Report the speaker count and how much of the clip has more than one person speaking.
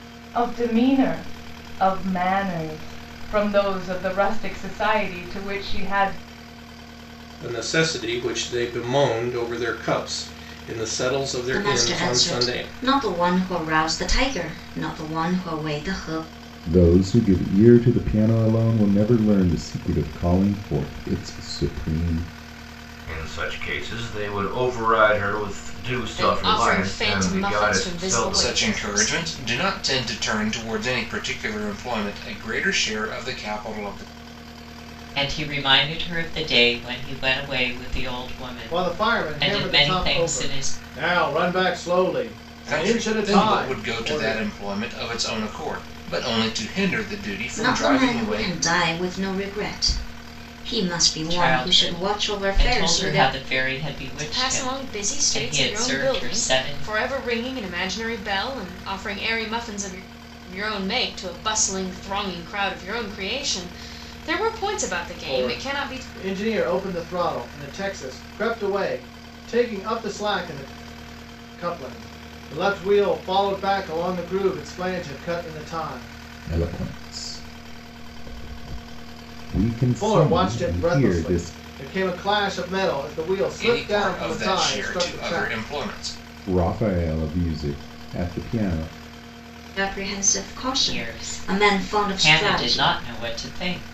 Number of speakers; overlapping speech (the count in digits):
9, about 22%